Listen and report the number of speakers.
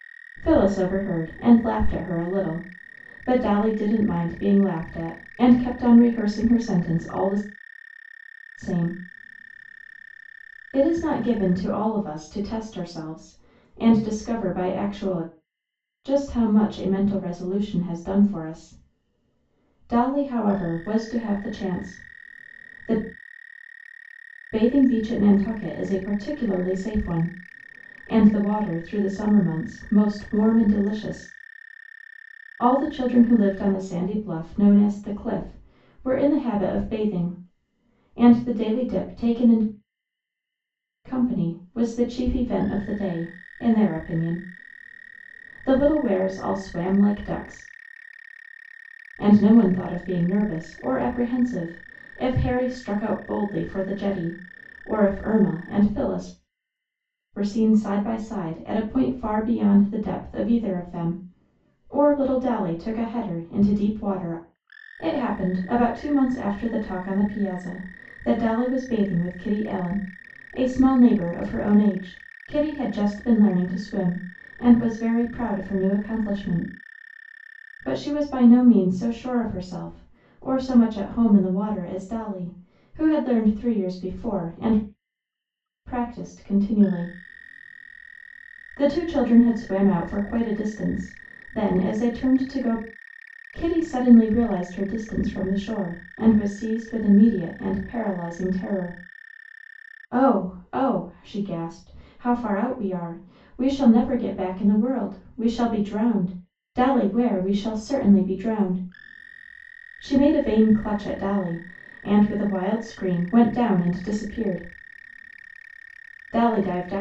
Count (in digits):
1